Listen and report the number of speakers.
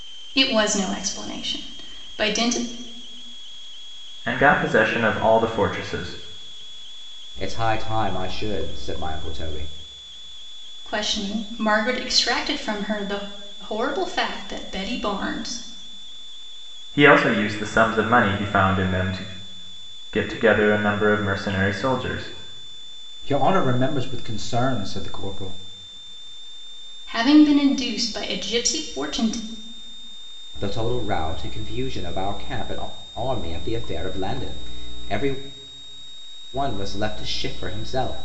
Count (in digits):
3